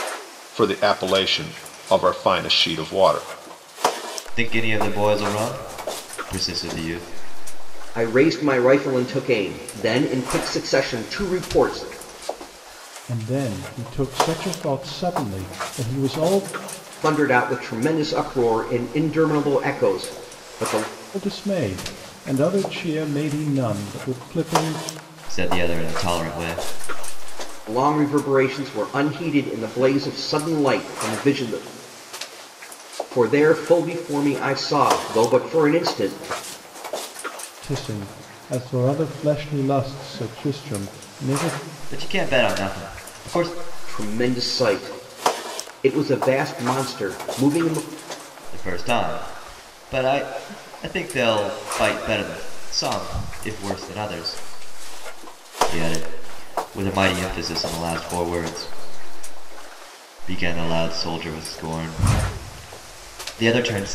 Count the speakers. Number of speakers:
four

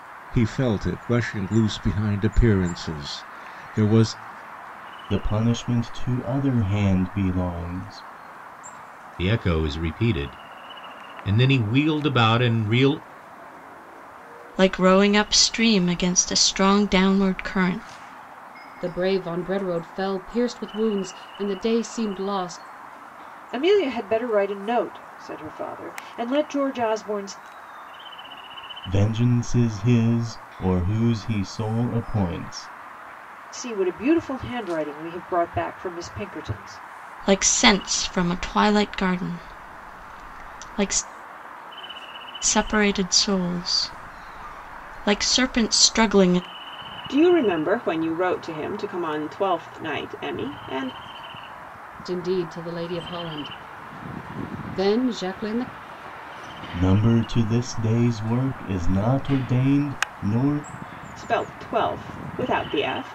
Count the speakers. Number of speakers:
six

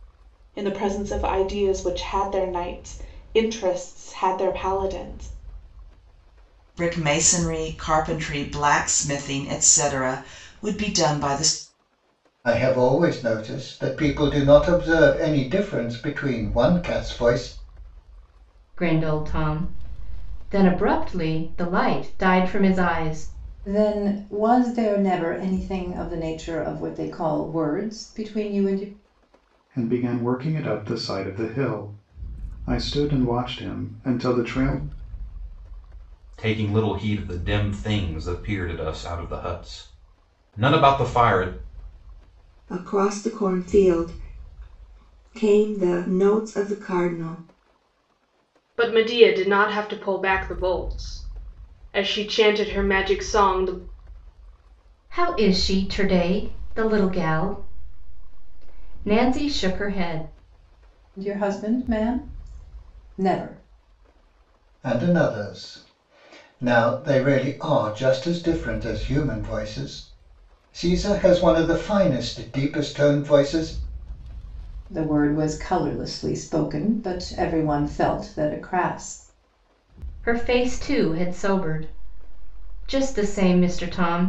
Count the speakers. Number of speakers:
nine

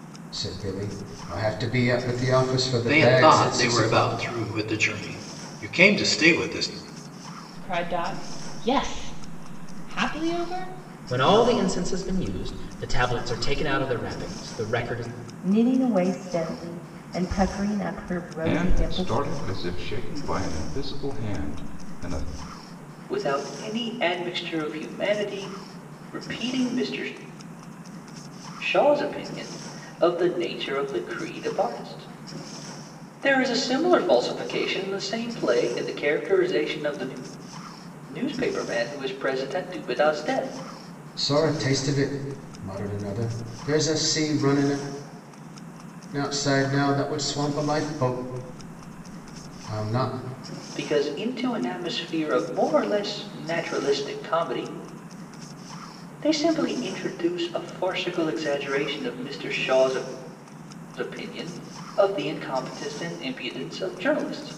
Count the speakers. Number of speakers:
seven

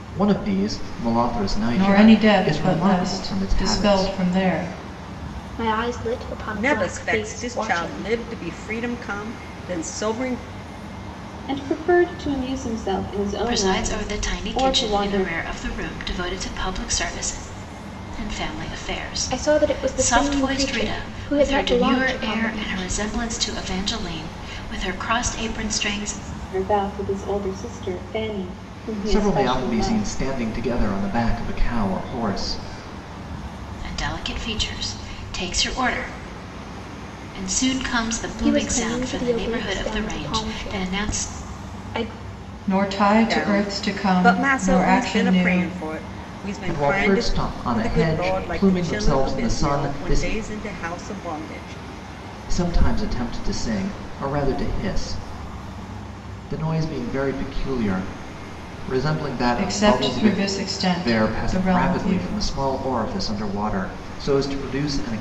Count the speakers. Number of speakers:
six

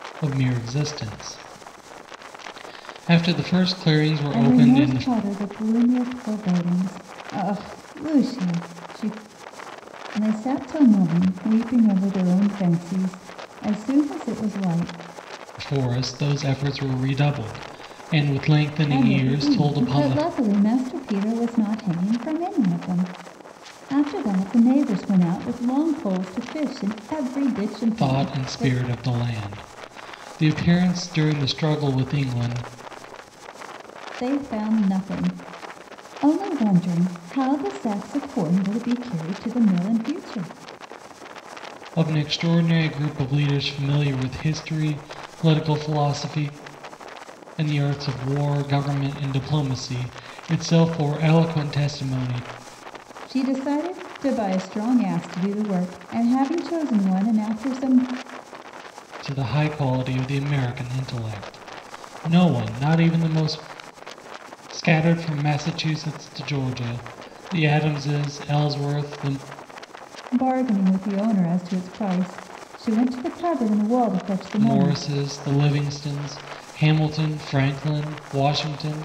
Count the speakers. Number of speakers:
two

